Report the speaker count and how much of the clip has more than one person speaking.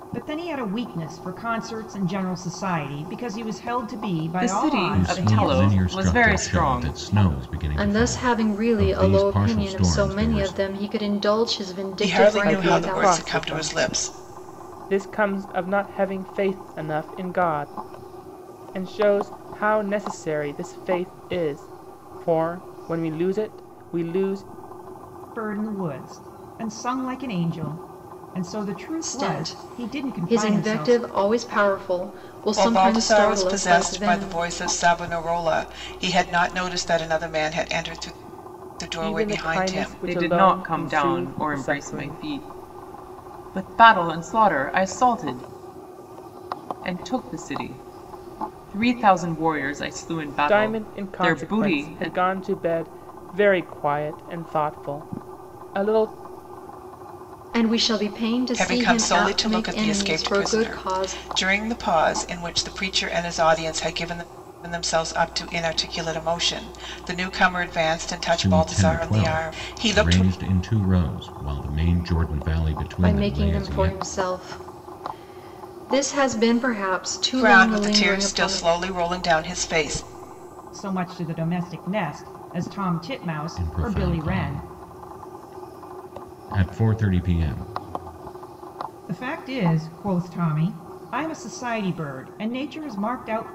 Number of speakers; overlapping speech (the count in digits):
6, about 27%